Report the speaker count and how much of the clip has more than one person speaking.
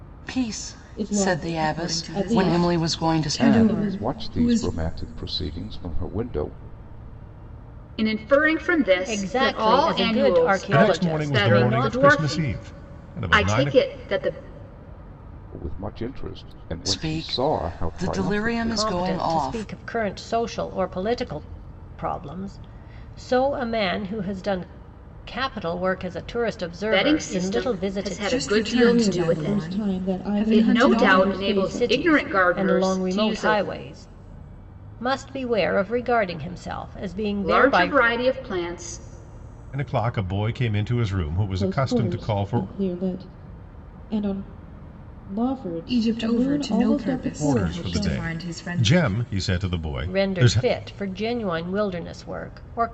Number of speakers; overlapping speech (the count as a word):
seven, about 44%